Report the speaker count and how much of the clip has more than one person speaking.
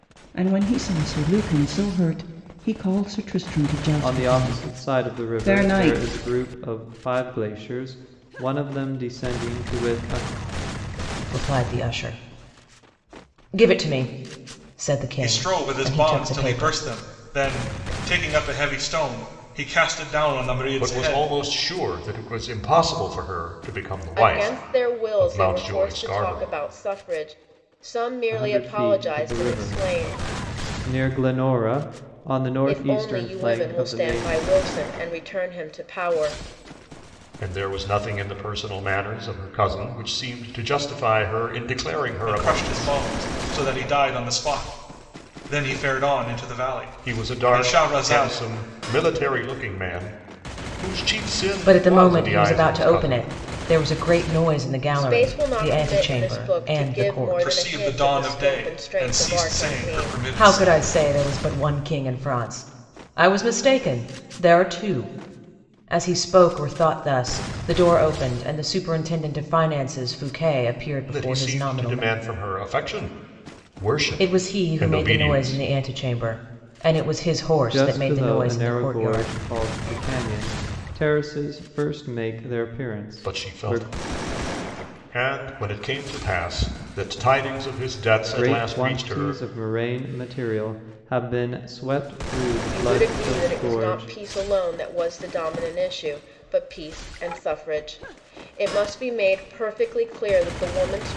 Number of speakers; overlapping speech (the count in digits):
6, about 27%